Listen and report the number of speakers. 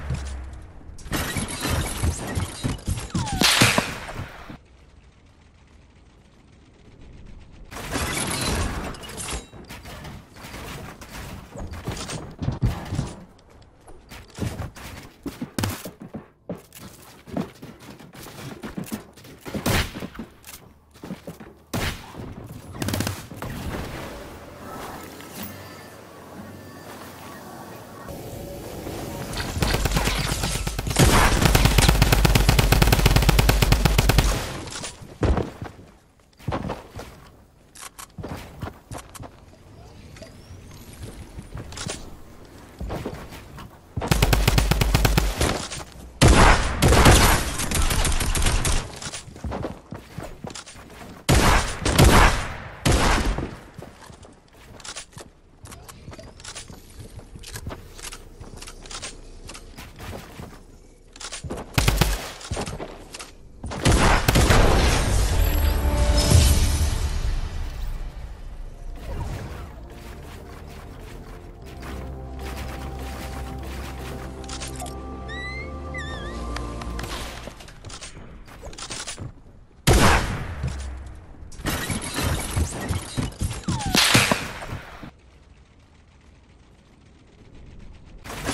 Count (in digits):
0